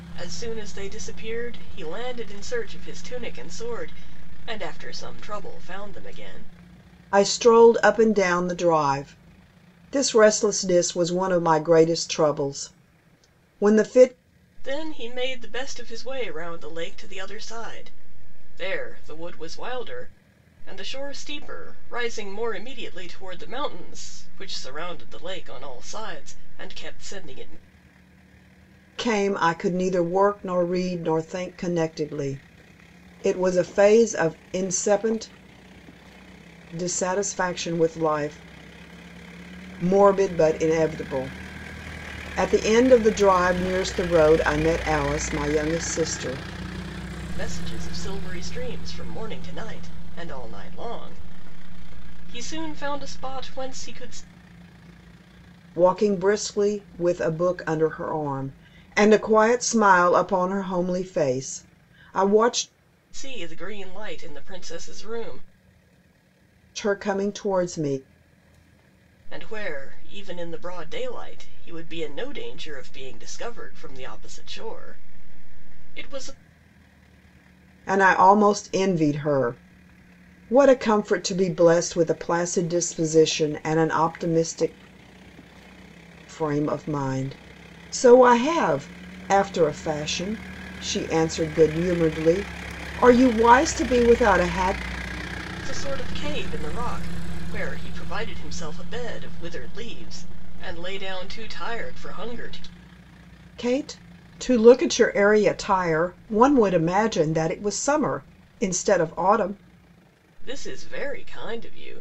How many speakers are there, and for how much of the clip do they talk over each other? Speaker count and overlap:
2, no overlap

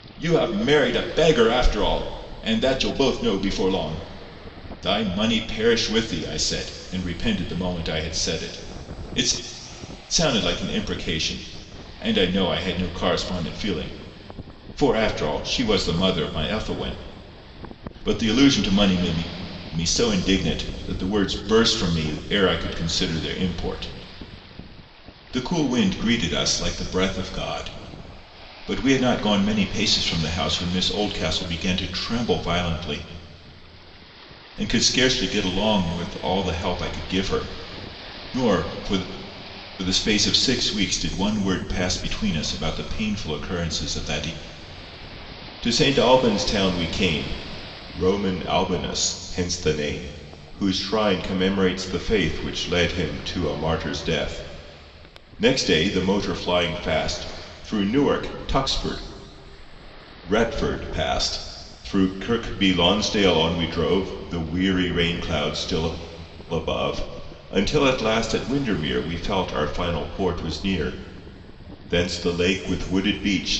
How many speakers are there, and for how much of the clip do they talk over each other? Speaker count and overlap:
1, no overlap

